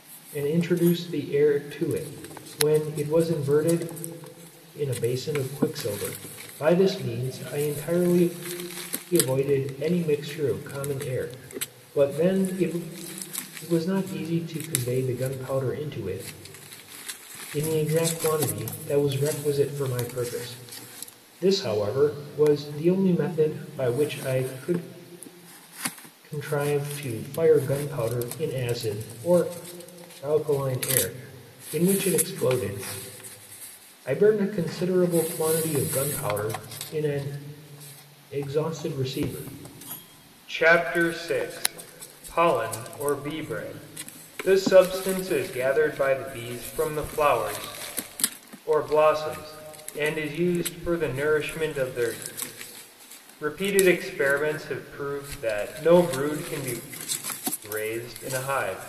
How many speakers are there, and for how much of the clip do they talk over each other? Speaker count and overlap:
one, no overlap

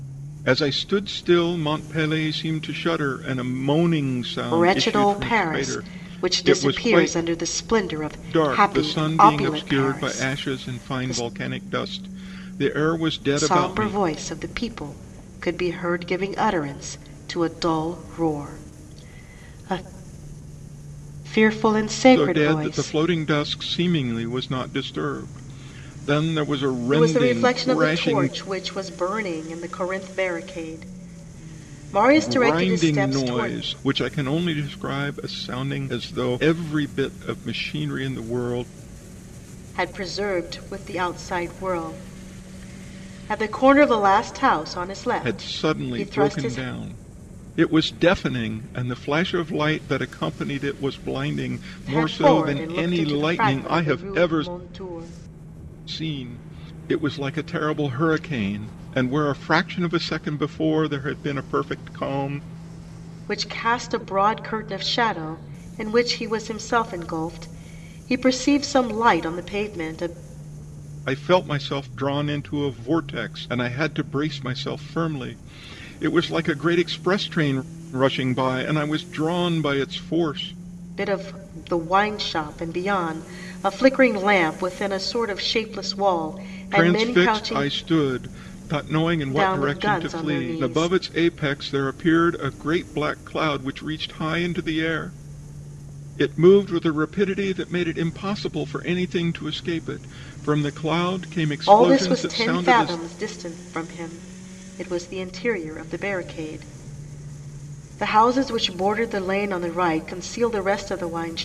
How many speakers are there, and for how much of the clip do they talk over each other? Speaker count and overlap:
two, about 17%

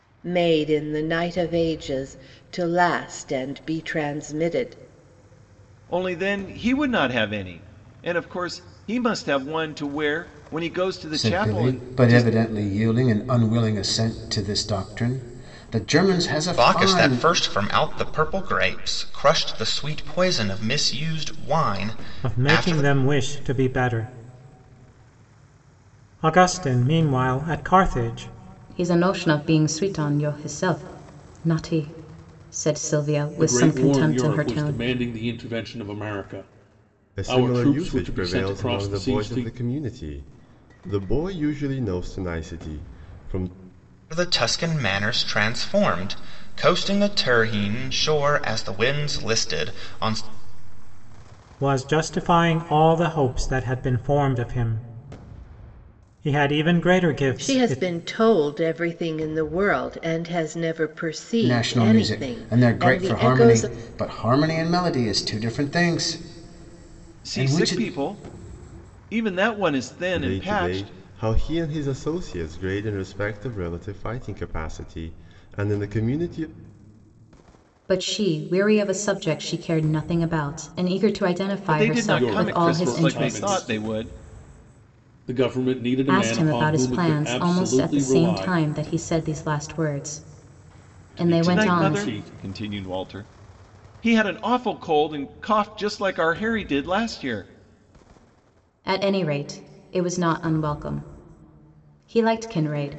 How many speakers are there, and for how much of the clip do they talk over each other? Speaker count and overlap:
eight, about 16%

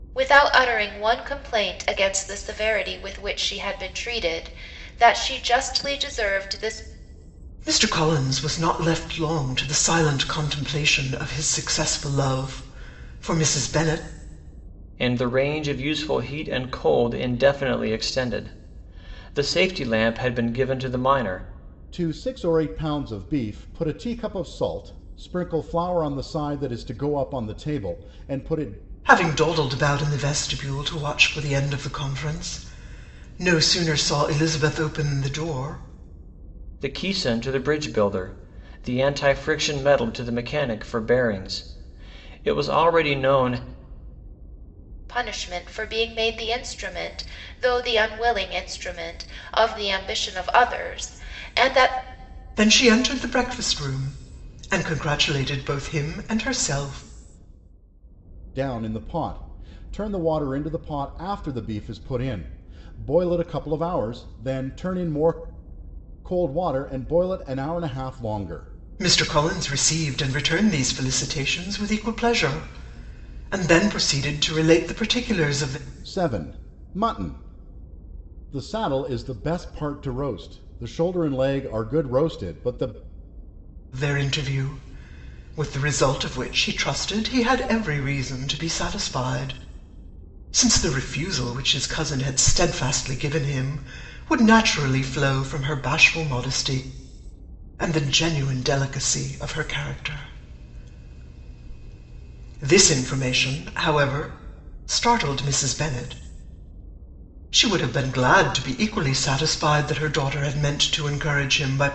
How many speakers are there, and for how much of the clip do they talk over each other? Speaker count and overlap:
four, no overlap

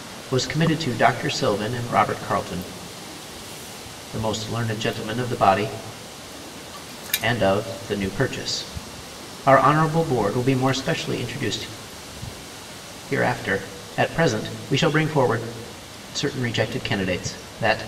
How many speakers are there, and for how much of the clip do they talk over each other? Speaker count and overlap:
one, no overlap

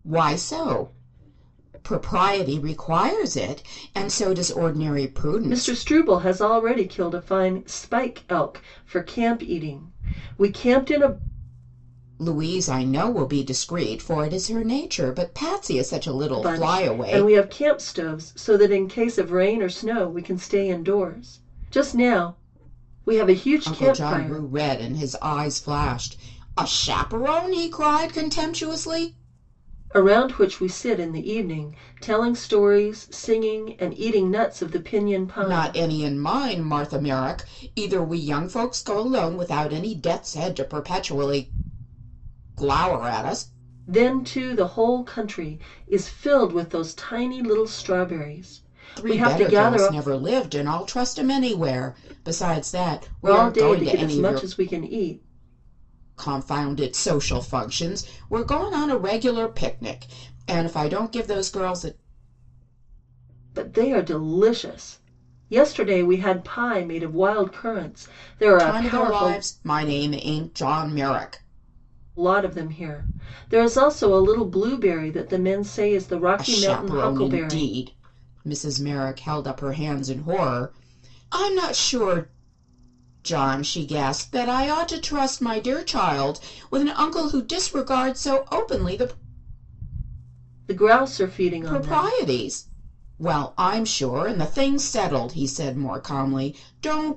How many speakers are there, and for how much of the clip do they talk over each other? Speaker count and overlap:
two, about 8%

